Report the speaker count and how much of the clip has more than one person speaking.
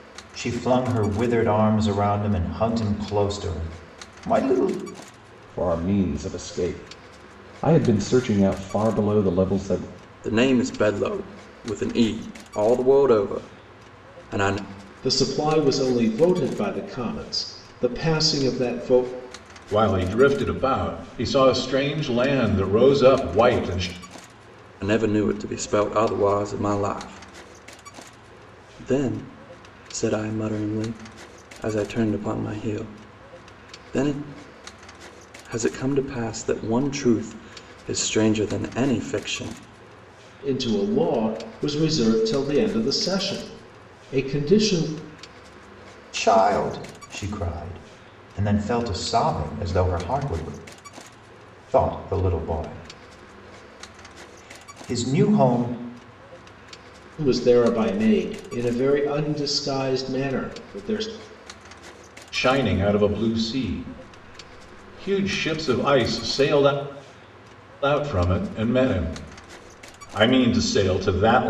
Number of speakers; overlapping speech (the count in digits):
5, no overlap